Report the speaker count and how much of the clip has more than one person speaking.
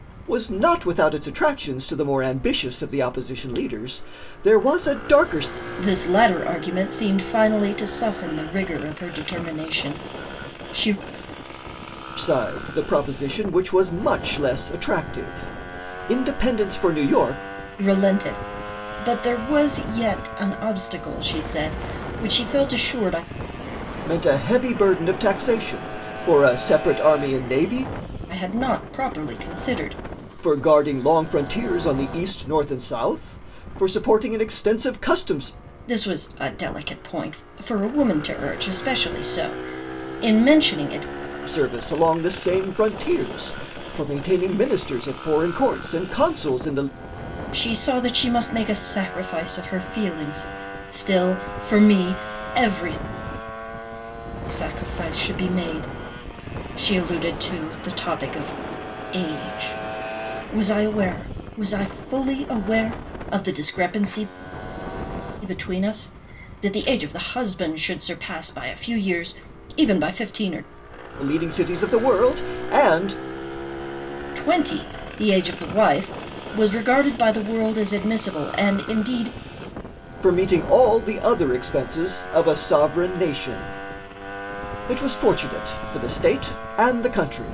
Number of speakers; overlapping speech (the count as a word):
two, no overlap